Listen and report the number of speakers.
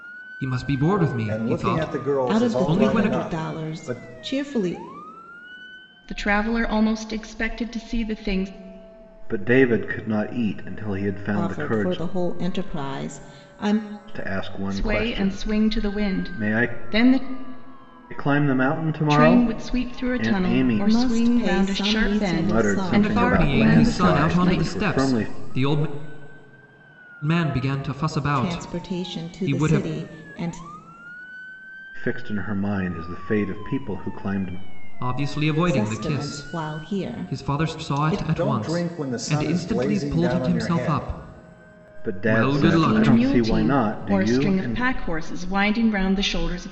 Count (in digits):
5